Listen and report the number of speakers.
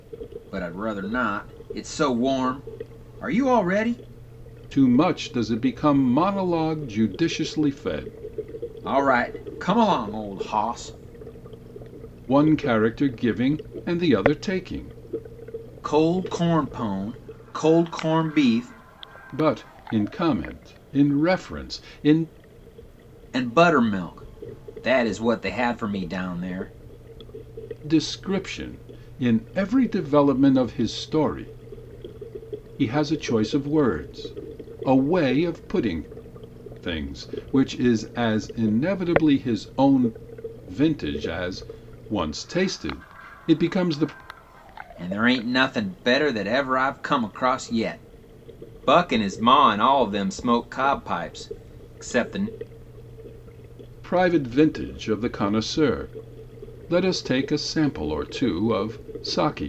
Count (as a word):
two